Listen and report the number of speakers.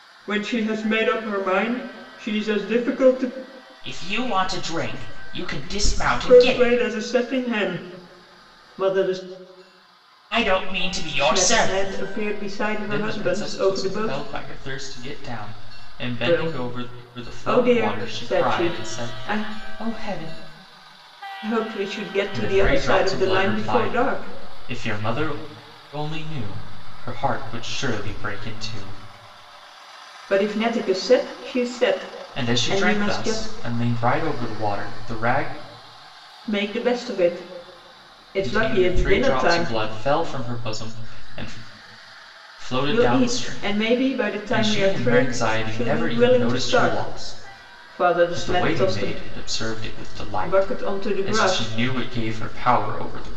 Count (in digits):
2